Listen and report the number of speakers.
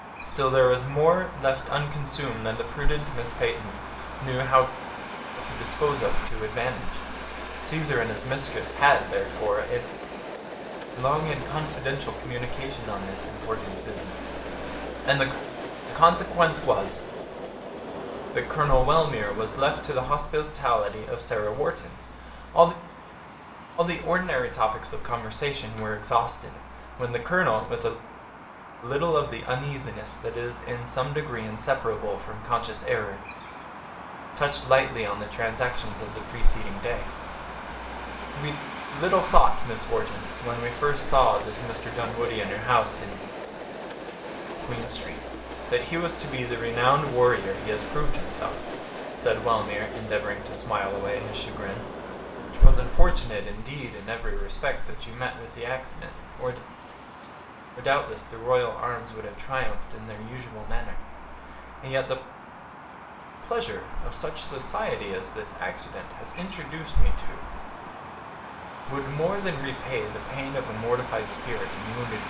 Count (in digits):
1